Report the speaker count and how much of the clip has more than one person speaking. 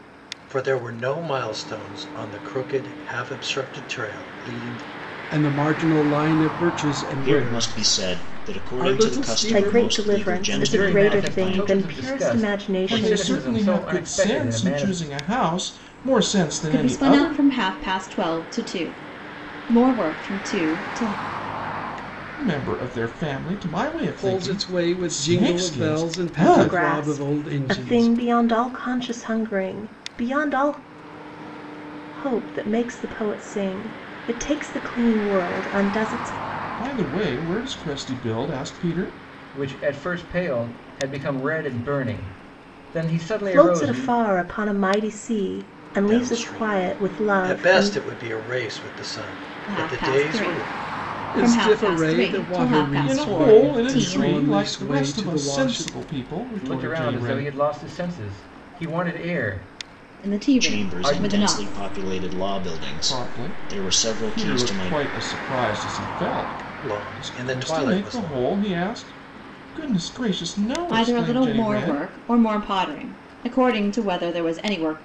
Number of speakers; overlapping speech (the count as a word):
seven, about 38%